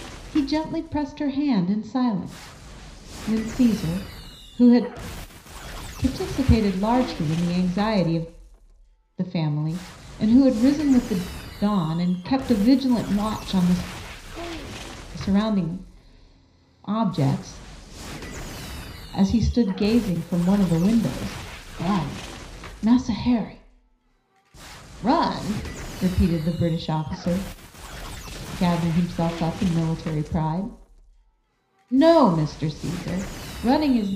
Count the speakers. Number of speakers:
1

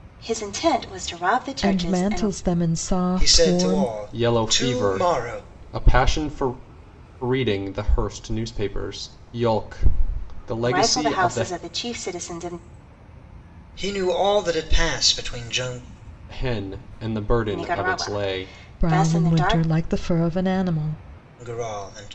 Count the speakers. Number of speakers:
4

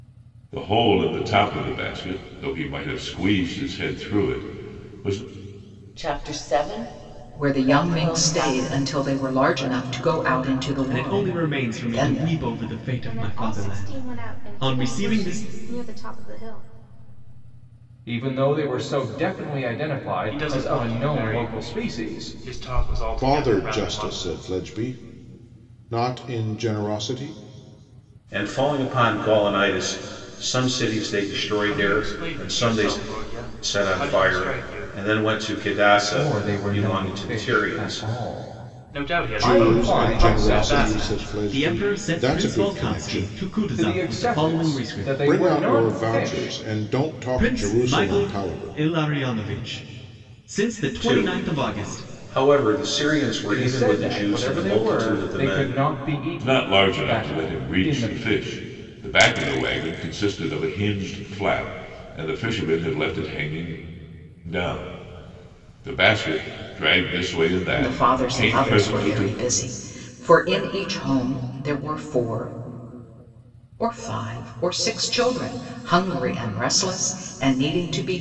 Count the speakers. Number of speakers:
9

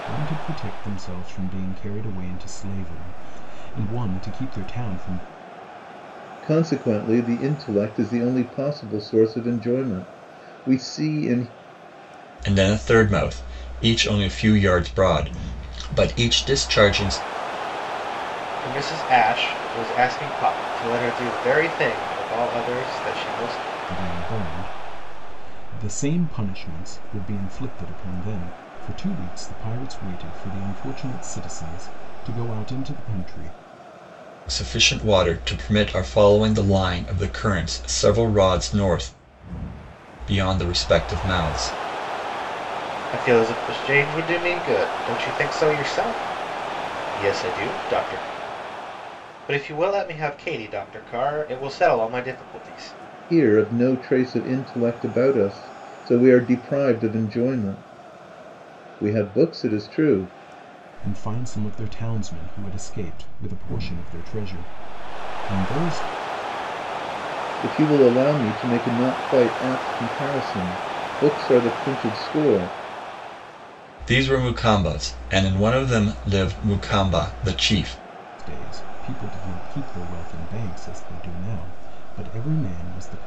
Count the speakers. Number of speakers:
4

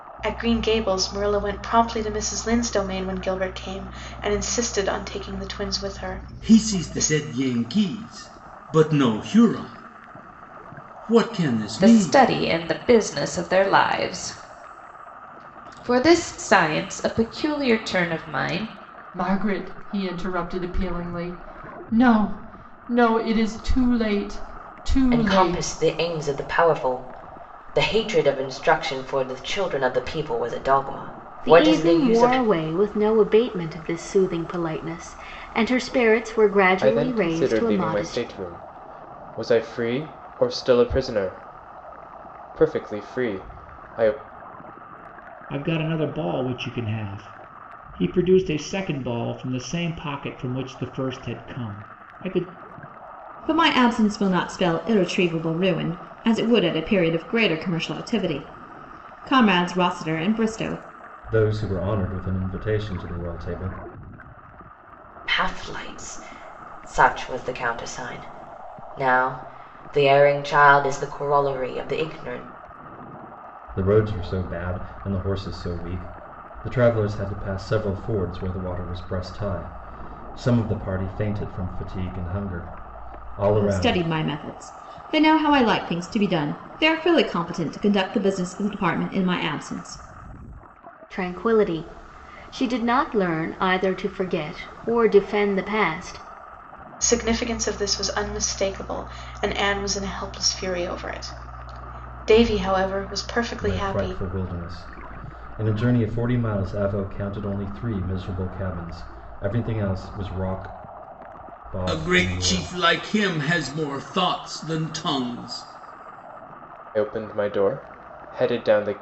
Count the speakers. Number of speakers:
10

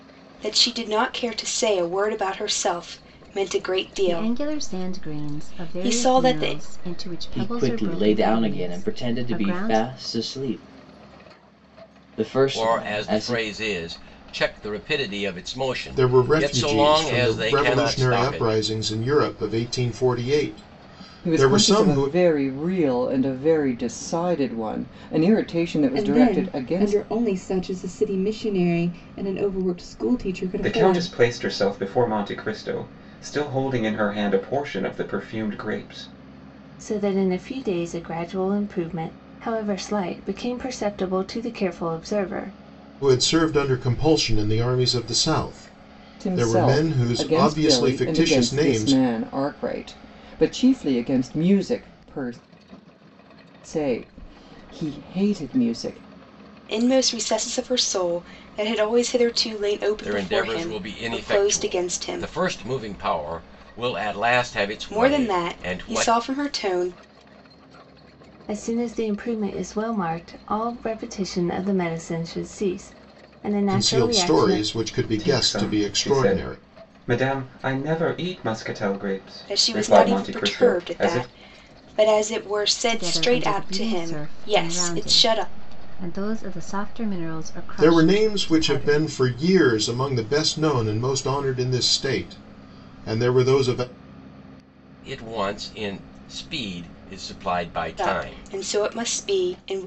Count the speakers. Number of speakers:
9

